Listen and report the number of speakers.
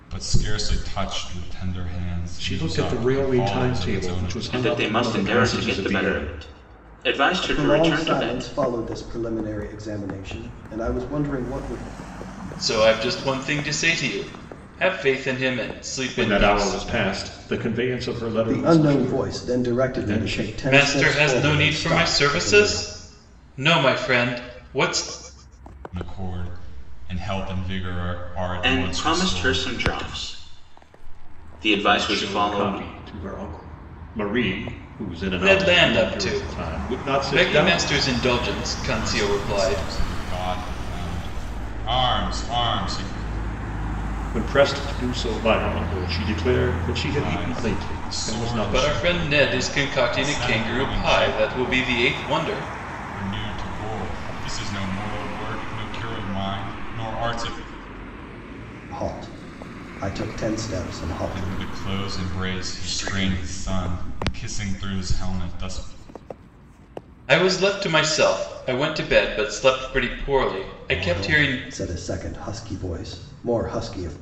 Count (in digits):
5